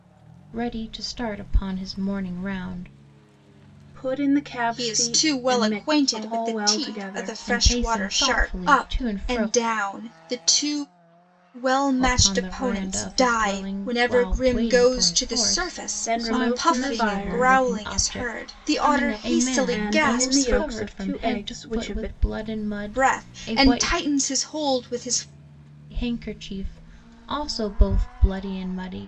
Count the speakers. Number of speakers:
3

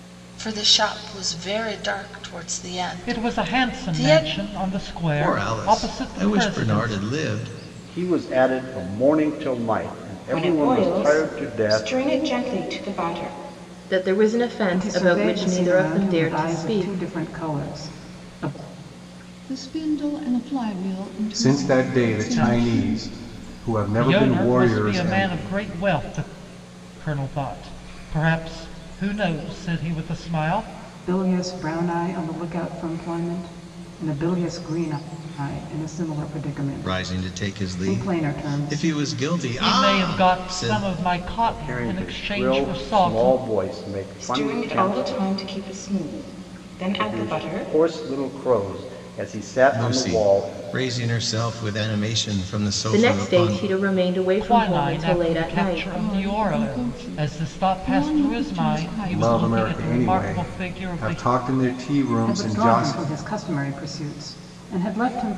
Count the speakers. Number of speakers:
9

